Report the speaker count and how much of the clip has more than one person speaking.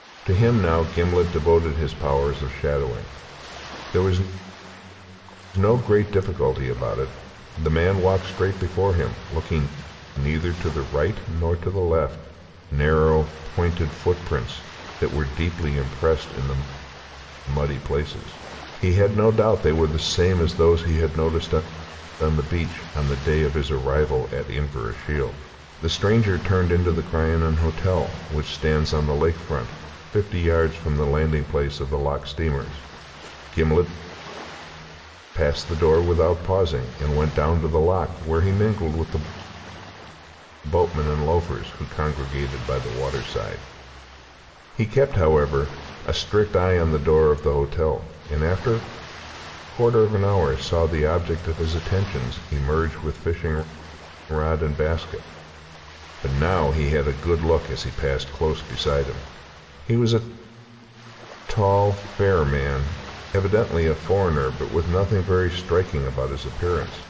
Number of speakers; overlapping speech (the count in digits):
1, no overlap